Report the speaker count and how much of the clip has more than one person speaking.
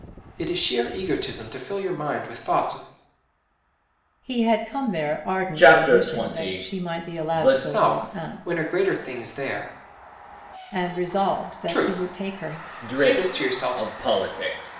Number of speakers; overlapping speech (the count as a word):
three, about 34%